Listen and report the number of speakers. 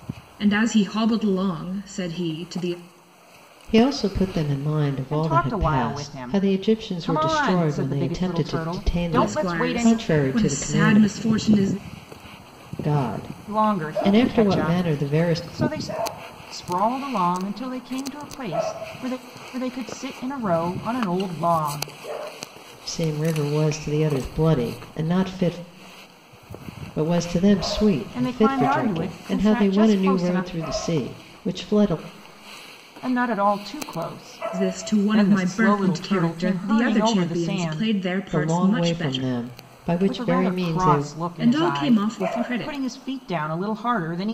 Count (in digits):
3